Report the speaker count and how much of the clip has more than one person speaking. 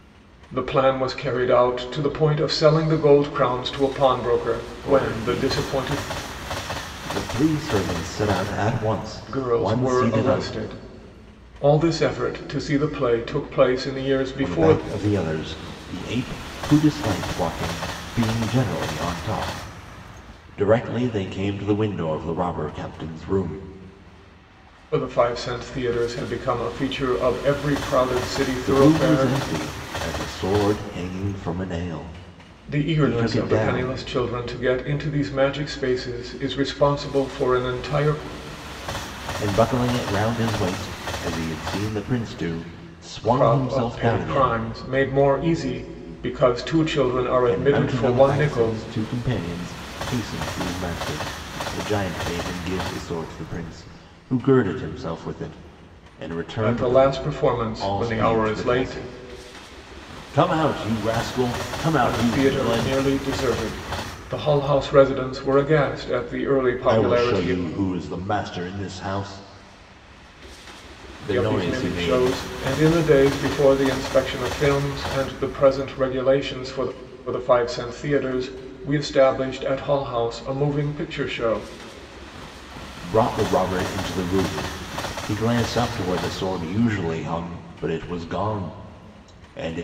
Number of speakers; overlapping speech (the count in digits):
2, about 13%